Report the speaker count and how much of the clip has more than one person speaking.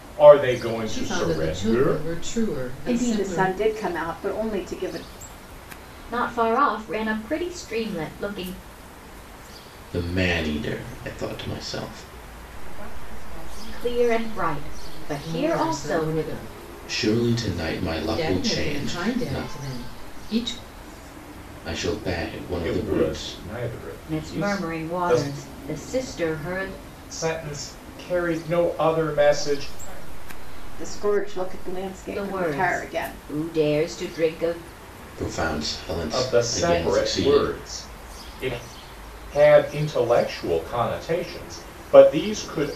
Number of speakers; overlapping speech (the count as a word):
six, about 28%